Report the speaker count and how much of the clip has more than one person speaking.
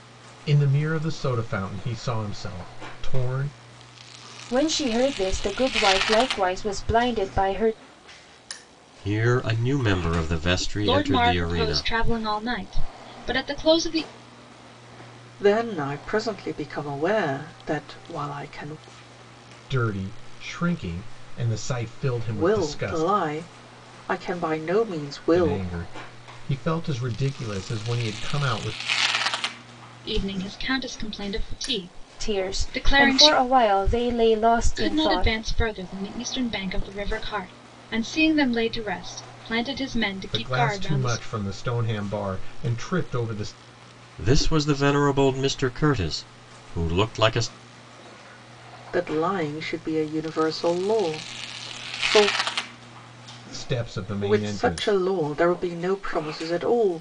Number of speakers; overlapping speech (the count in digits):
5, about 10%